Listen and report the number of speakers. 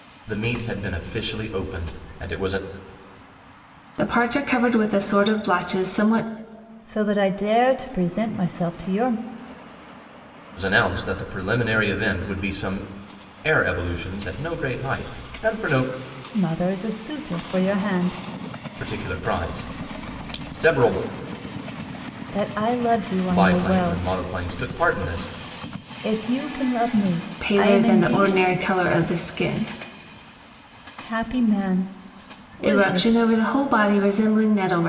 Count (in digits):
3